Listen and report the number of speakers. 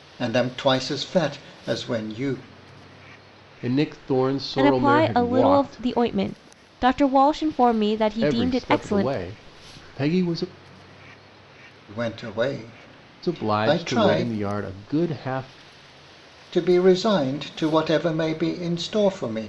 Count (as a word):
three